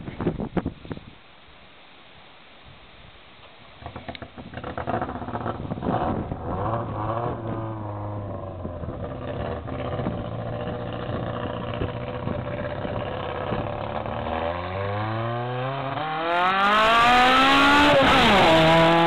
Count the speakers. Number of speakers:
zero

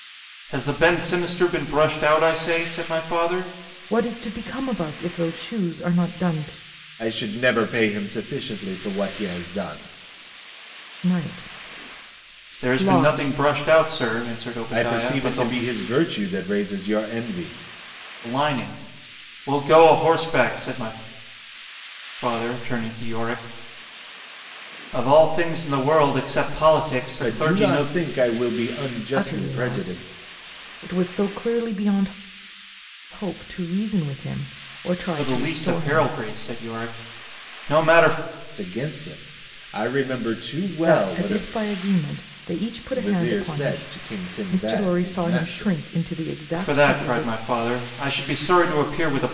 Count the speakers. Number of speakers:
three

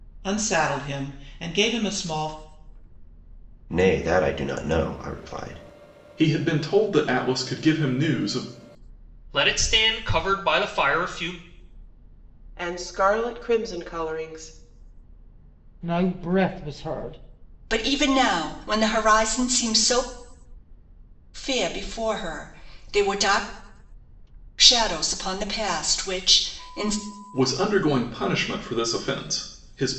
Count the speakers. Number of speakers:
seven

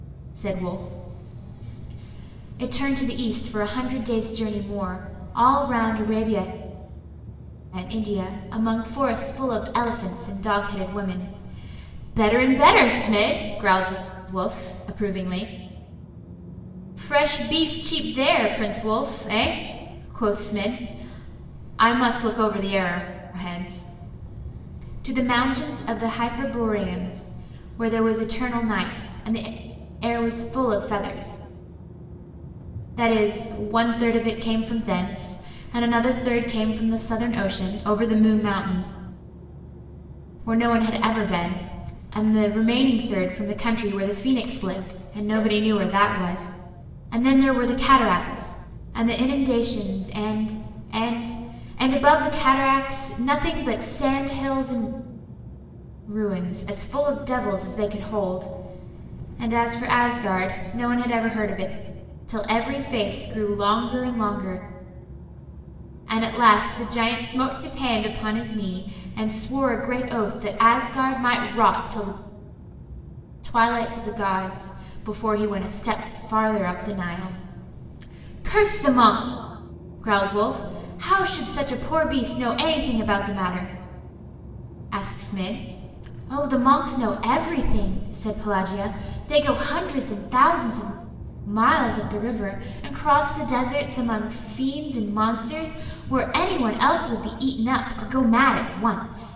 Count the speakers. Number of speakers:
one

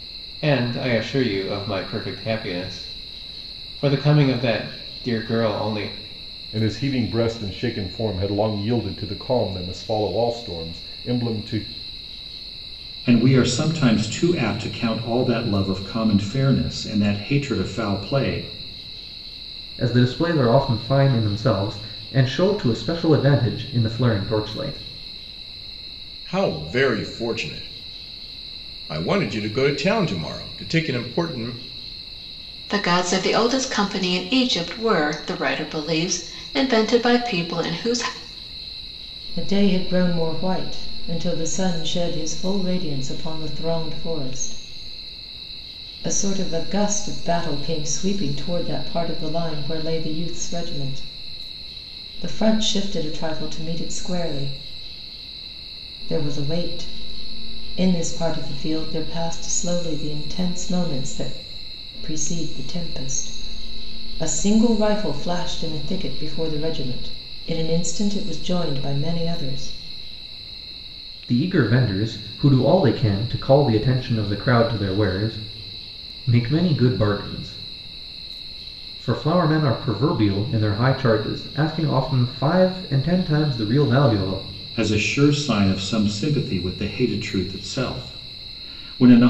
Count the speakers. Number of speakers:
seven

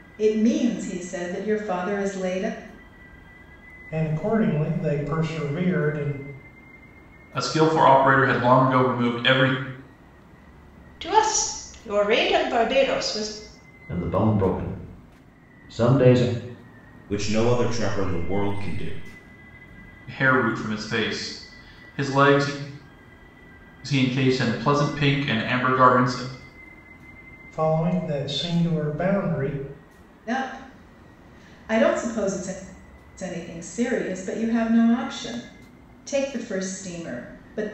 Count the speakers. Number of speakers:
six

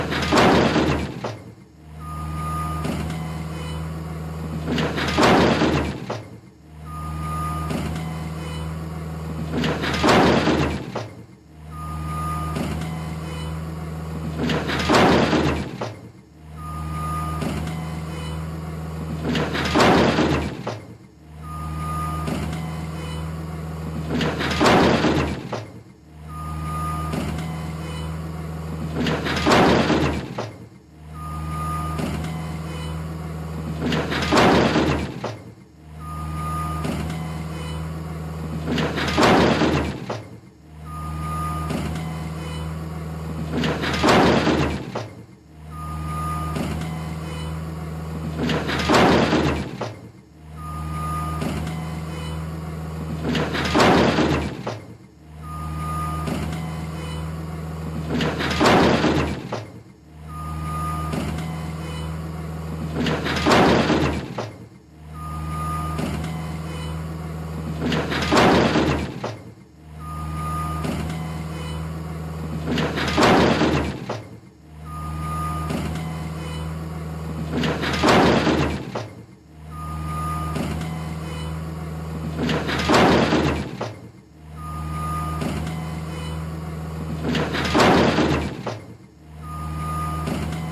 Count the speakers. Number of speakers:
zero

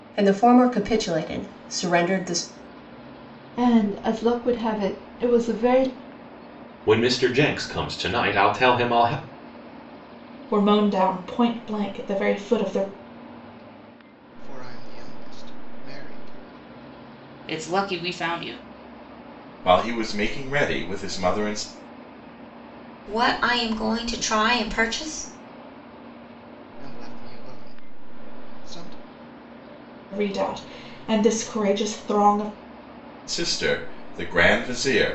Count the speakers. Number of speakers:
eight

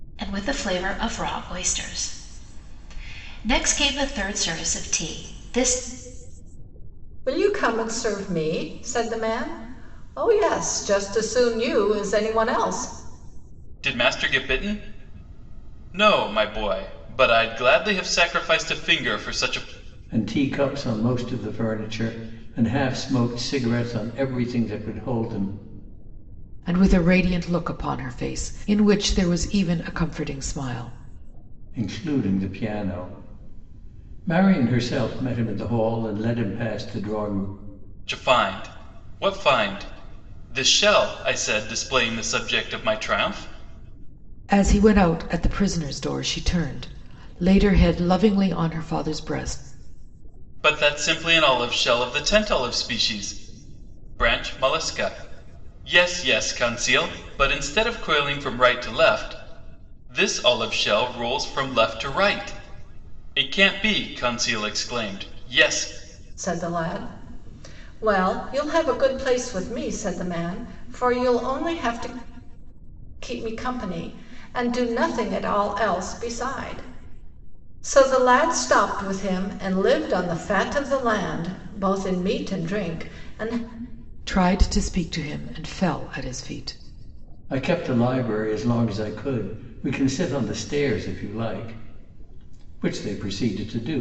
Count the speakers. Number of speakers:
five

